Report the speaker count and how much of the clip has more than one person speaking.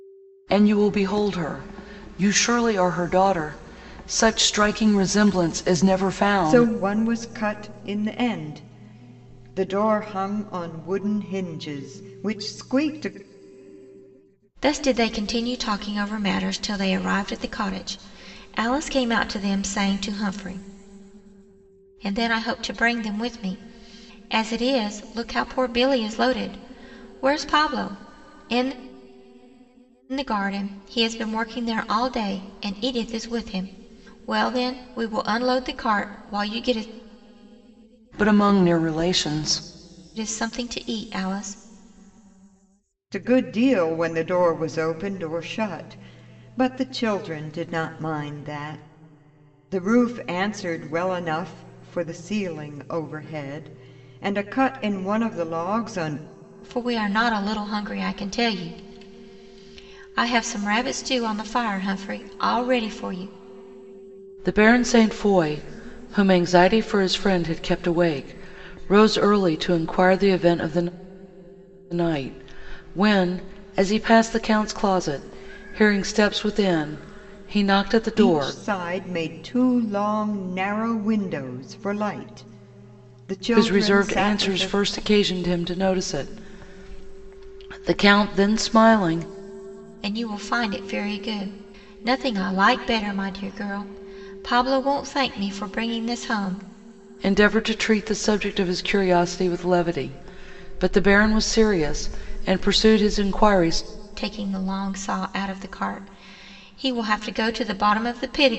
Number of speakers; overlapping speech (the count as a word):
three, about 2%